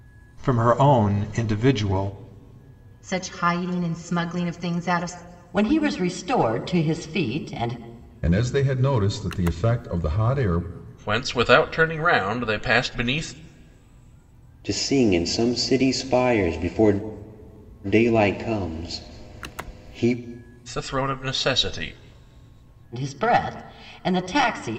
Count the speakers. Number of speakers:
six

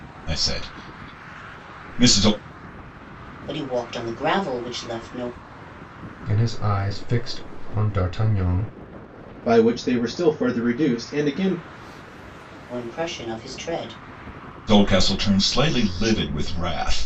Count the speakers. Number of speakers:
four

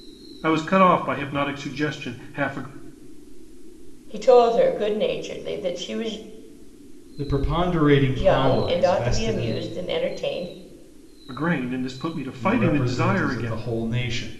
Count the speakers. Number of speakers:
three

